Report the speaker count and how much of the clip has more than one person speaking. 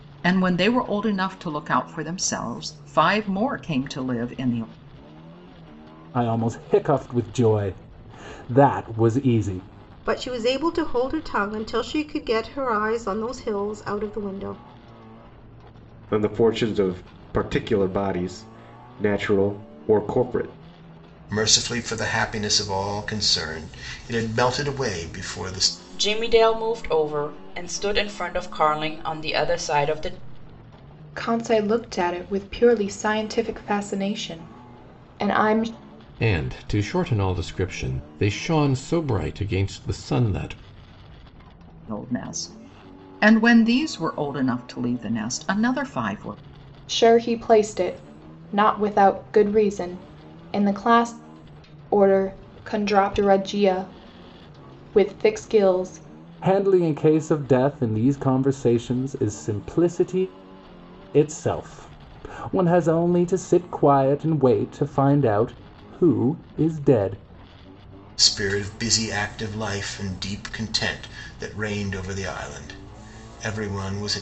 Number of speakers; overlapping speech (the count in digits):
8, no overlap